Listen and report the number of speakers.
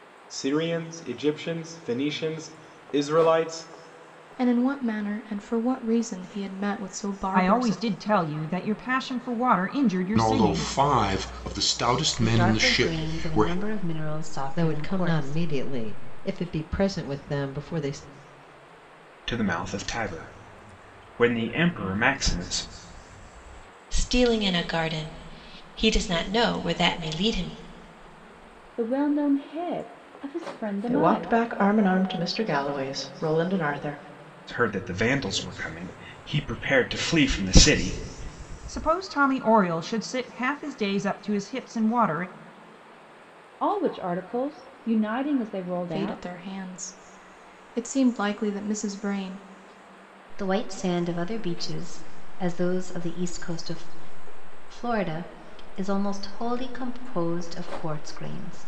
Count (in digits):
10